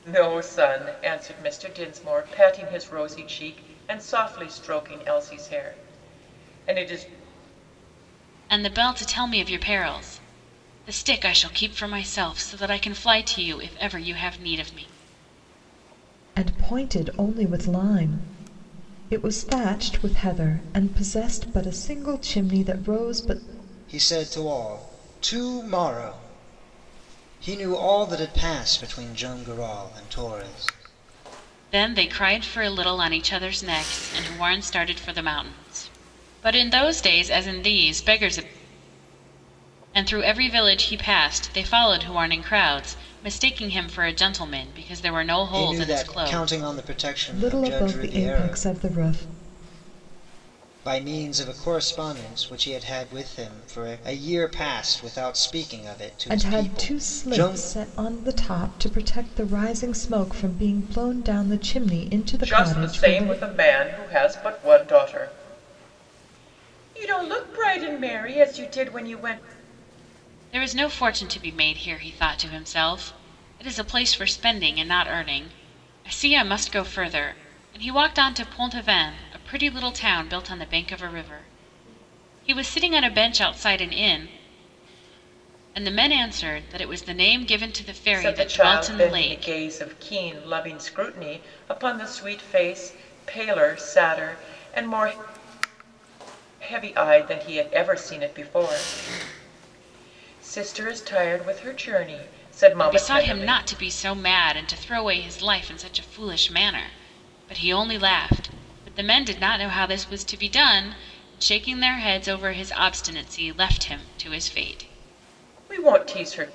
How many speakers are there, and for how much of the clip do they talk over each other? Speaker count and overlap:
4, about 6%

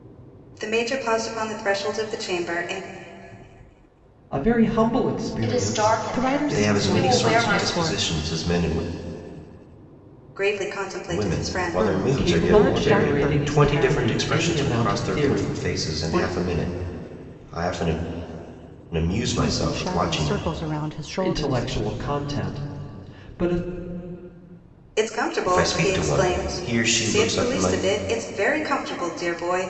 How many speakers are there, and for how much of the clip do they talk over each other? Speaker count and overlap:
5, about 41%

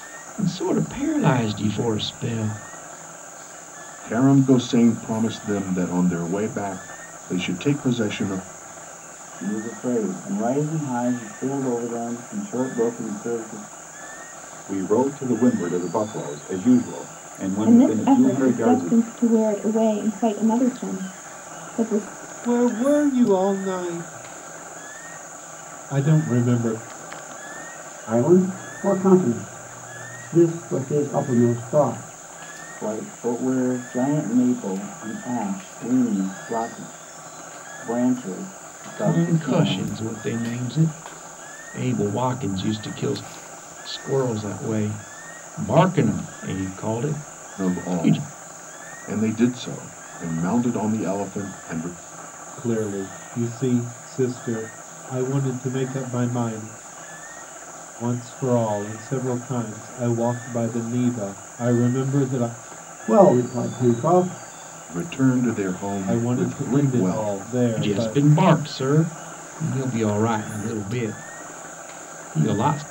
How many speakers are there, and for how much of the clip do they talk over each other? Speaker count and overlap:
7, about 7%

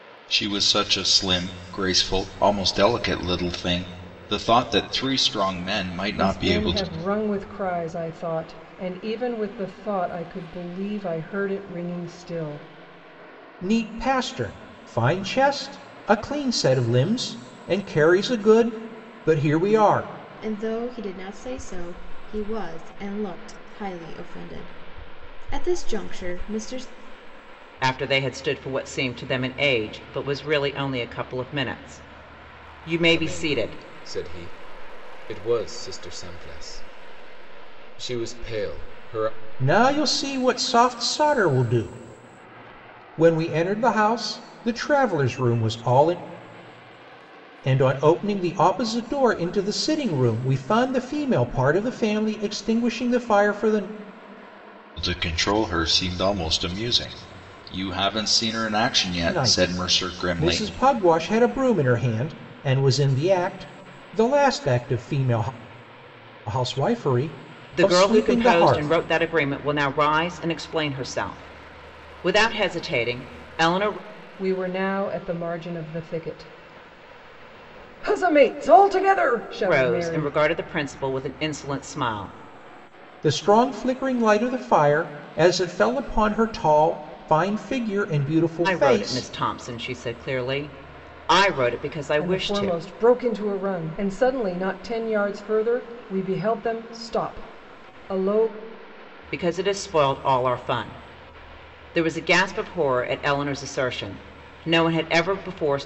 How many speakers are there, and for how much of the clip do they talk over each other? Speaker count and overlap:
6, about 6%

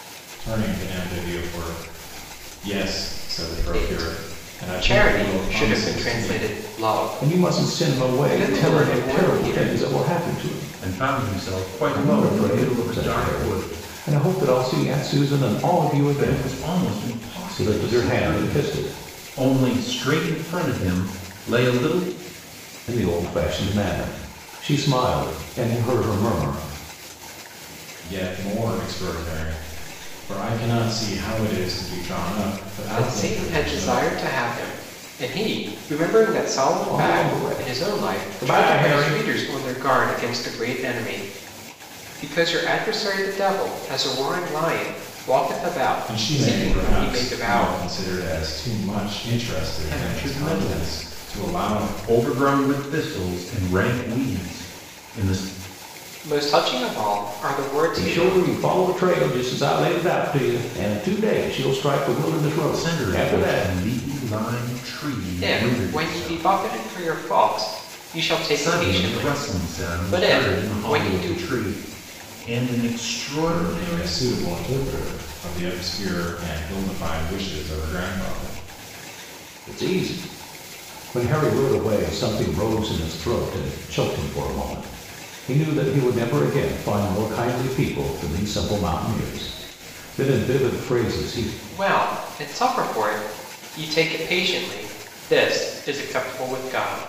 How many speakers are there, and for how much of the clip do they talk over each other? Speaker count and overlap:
4, about 26%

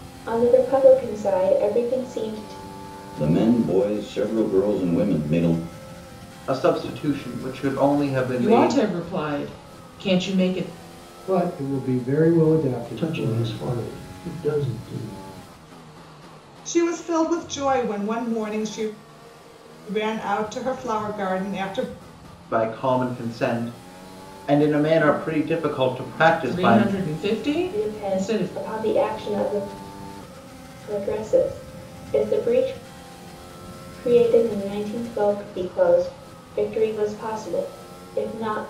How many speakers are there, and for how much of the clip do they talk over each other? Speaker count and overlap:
7, about 6%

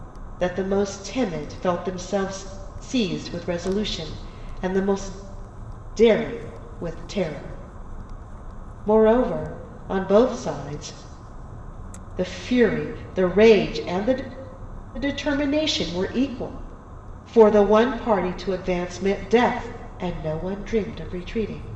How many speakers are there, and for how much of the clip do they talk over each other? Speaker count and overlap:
1, no overlap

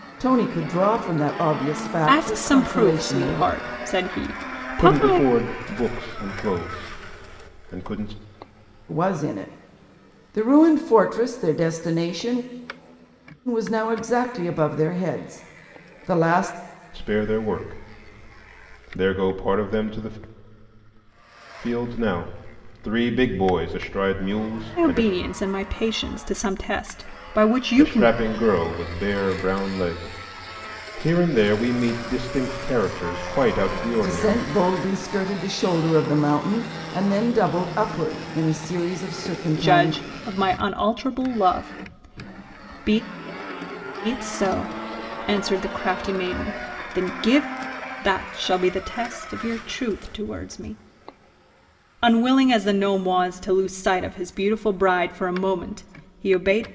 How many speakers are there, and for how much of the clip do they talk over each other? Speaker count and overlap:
3, about 6%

